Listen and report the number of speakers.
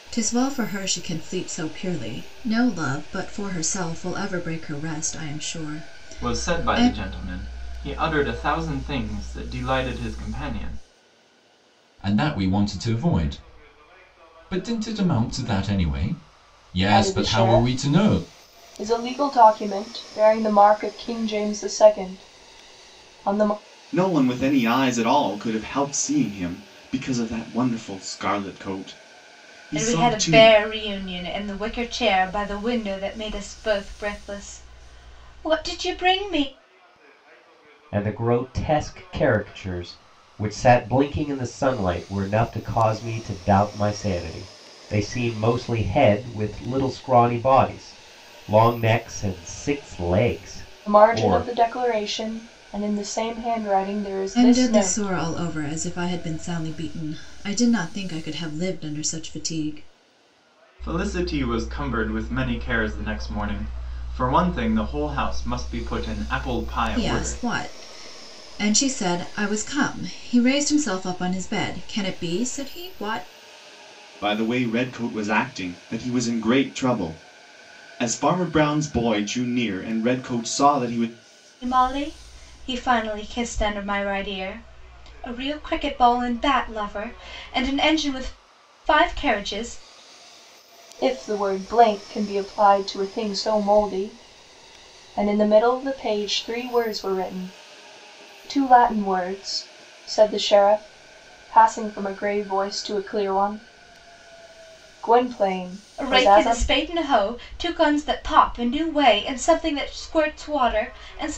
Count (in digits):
7